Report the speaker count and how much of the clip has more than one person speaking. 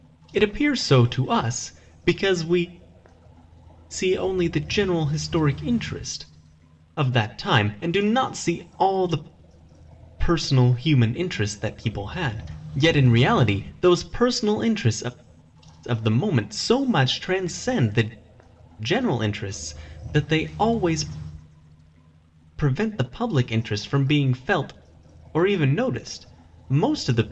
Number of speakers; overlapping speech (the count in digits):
1, no overlap